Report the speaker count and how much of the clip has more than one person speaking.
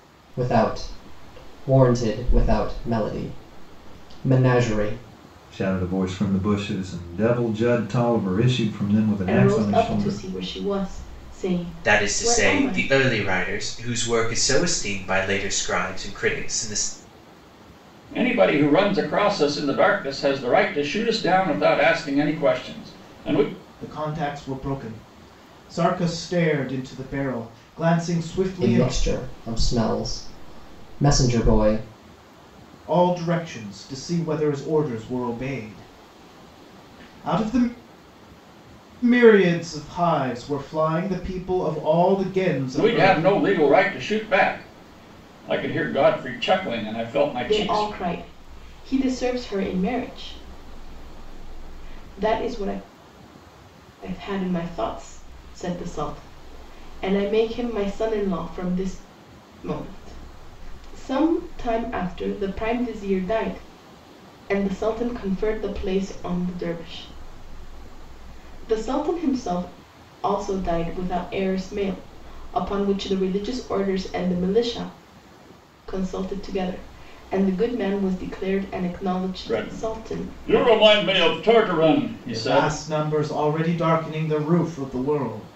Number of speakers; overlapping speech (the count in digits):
6, about 6%